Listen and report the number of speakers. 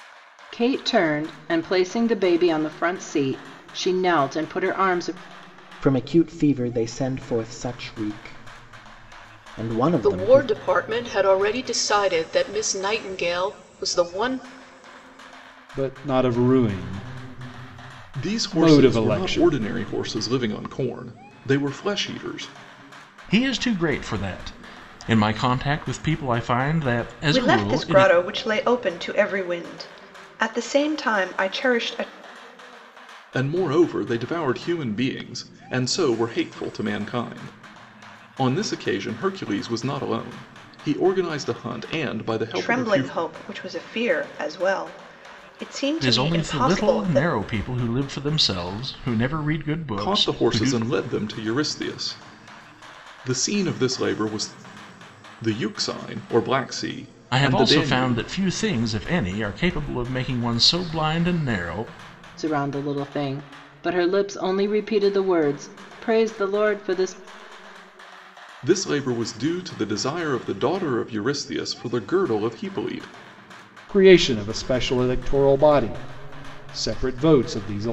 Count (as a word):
seven